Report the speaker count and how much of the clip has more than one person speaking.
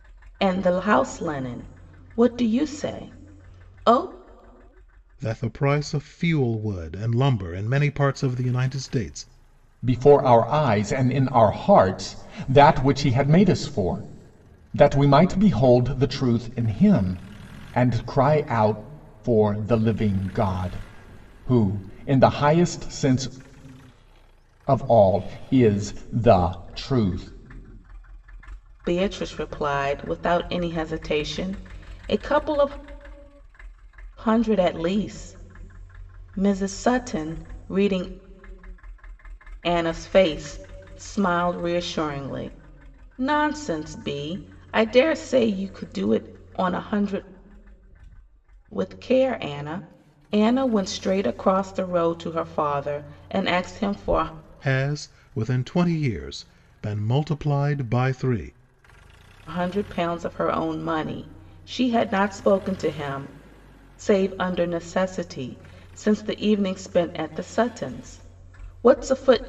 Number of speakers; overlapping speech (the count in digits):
3, no overlap